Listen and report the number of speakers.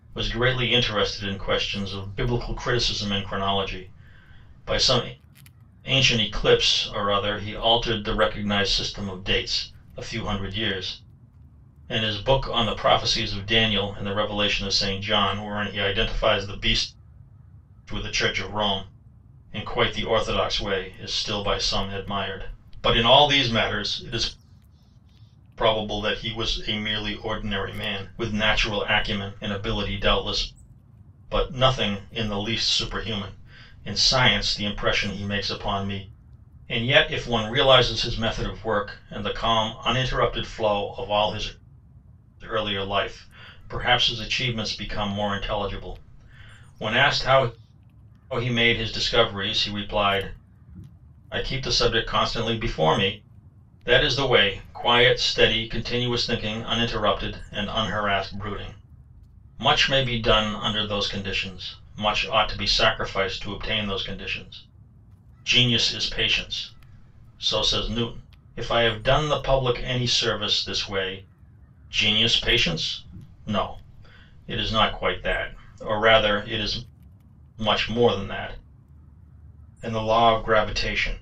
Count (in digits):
1